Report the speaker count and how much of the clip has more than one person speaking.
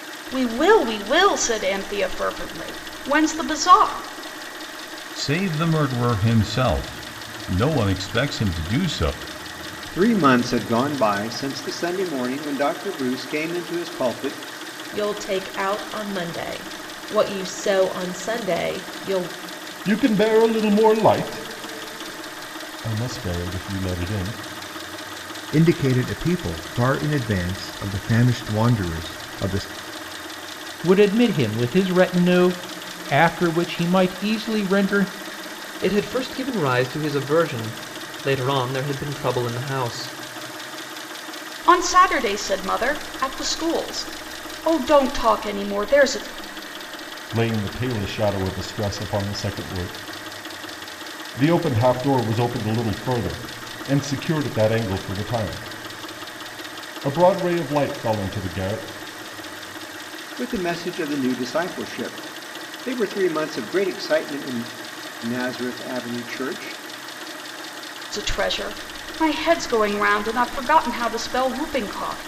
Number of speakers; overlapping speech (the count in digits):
8, no overlap